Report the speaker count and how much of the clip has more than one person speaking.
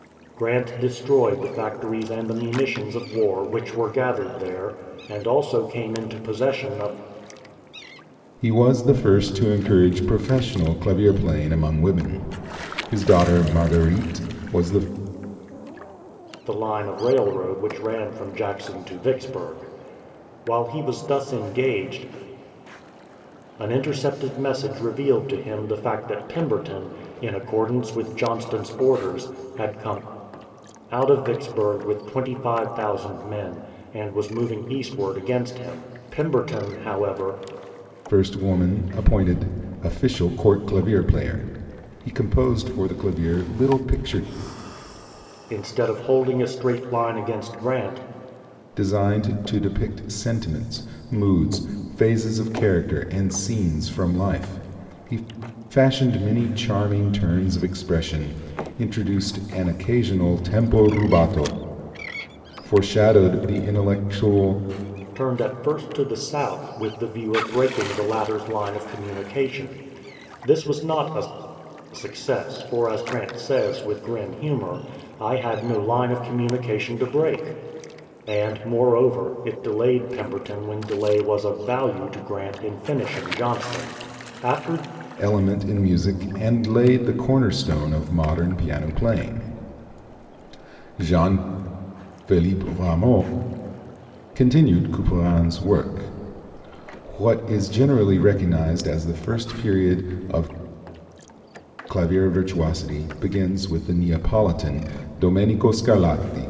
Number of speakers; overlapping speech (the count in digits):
2, no overlap